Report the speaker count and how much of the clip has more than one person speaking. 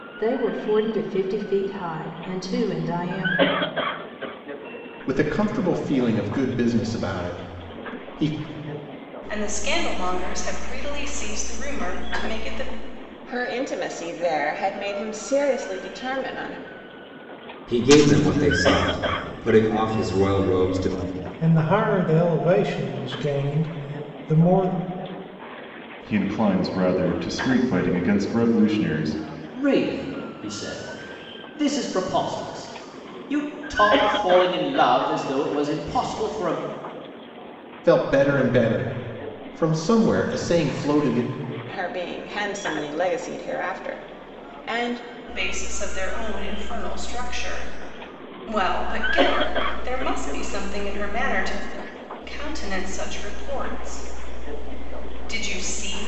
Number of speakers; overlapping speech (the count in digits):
8, no overlap